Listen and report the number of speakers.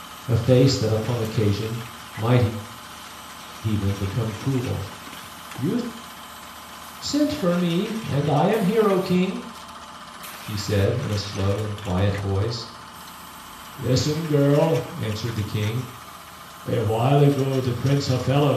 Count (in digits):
1